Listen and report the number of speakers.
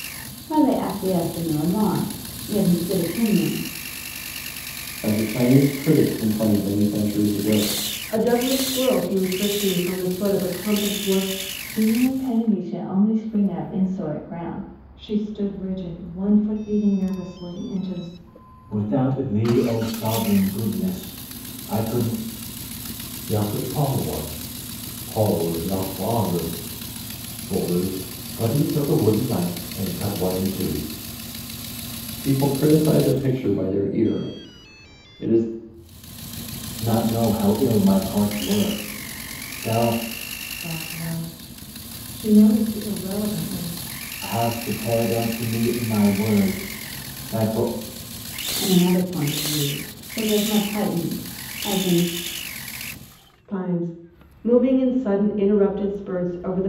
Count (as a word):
seven